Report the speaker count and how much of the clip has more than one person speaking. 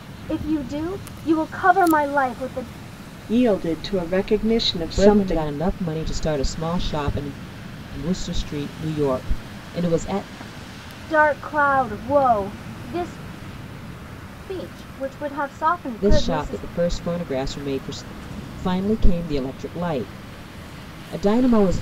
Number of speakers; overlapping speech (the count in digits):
3, about 6%